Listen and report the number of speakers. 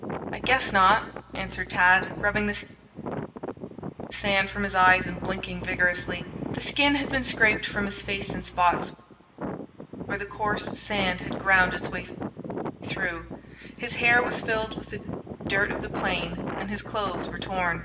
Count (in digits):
1